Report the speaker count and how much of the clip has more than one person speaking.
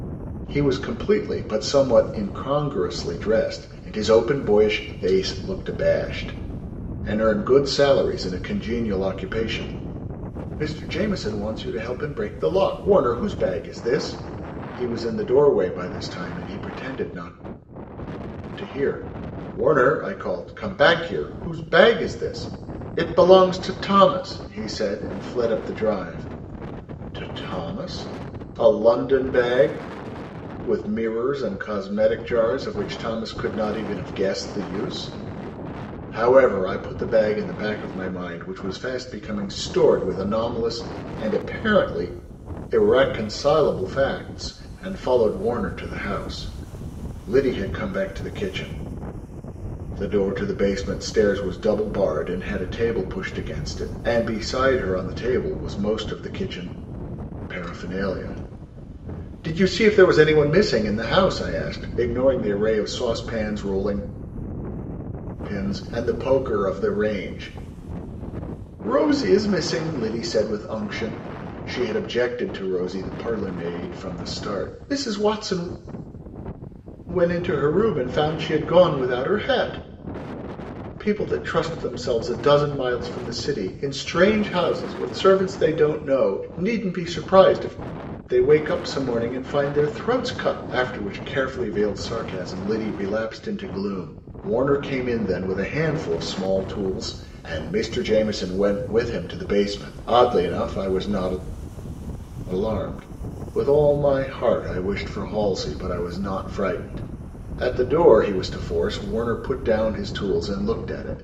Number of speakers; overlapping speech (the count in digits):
1, no overlap